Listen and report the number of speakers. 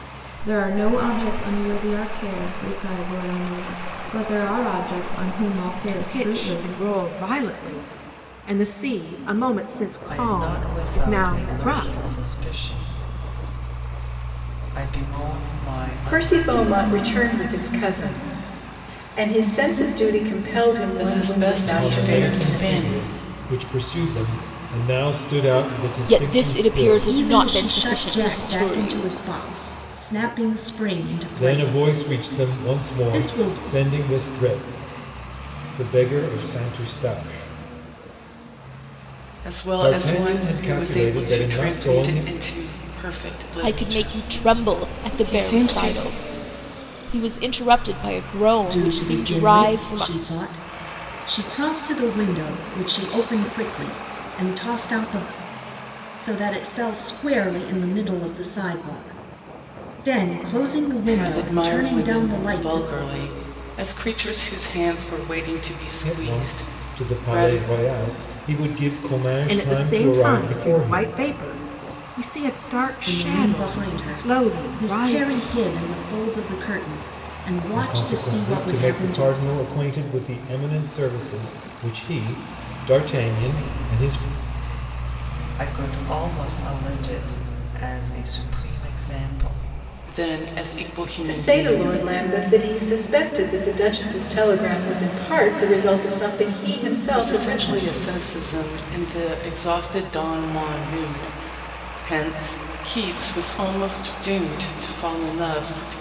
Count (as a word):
eight